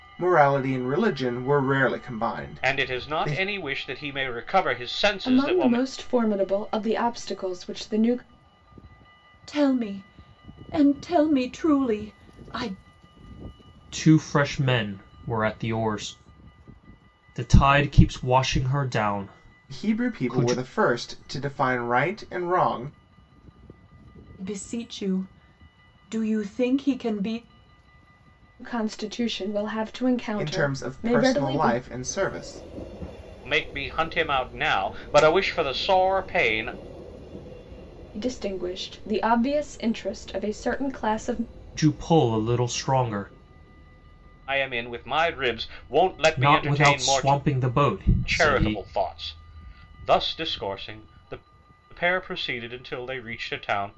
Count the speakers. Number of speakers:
five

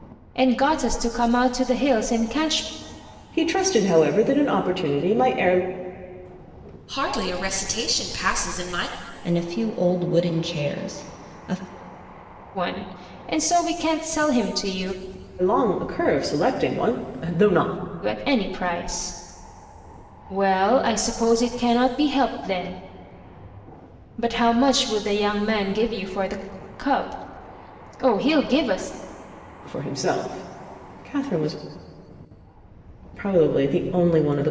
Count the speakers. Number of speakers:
four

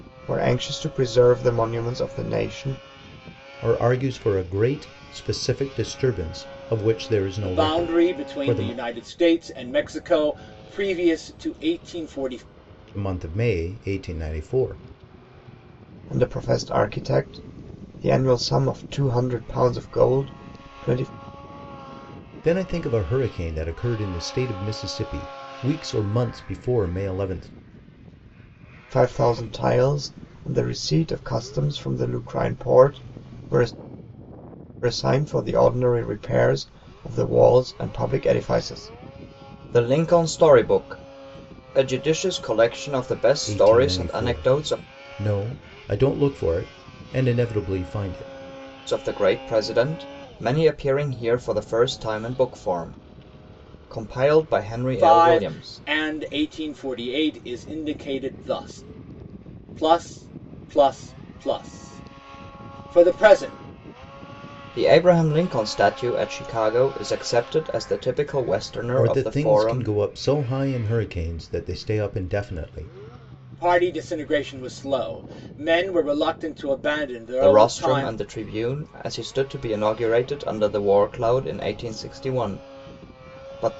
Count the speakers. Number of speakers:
three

